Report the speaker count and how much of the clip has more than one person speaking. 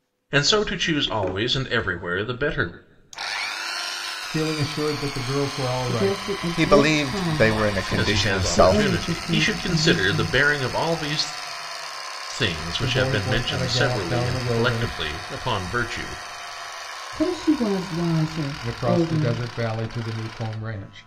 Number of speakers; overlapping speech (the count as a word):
four, about 35%